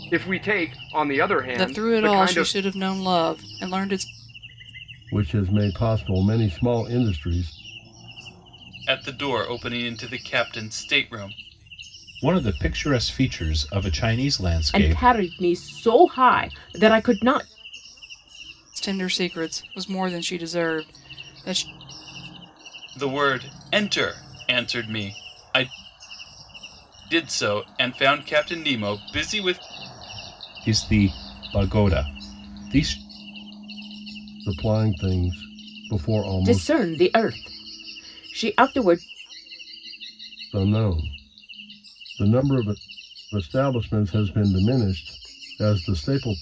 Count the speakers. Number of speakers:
six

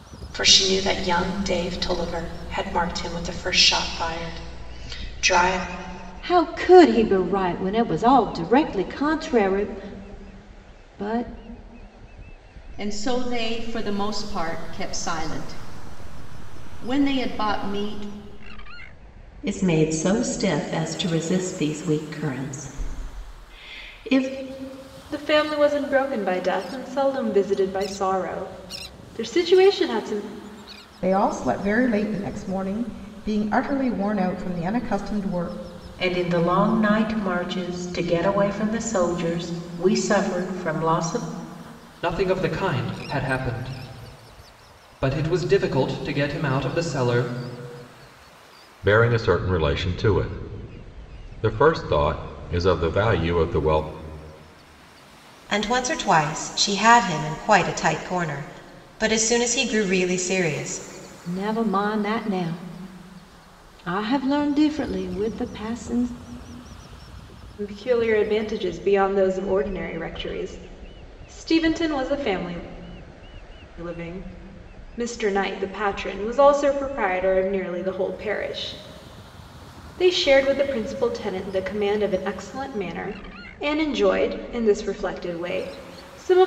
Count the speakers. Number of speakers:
ten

